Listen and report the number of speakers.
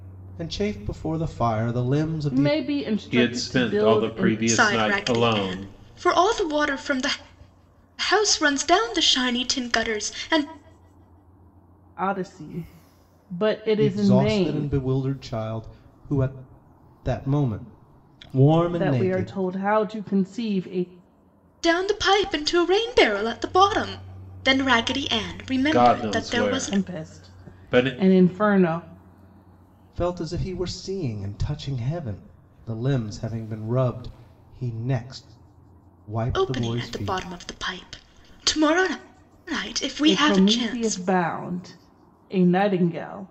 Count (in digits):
4